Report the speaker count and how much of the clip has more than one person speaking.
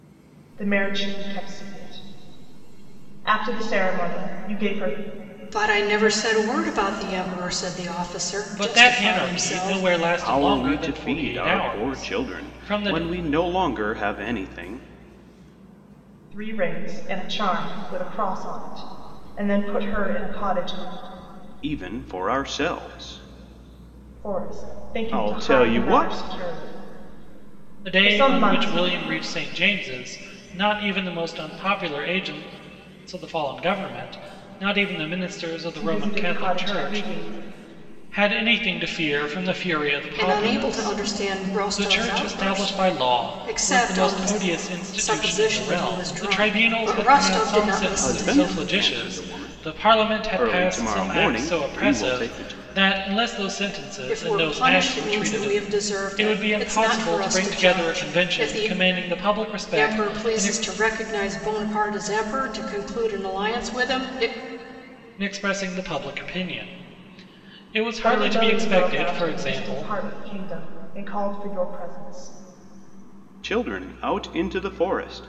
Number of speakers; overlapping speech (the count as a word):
four, about 35%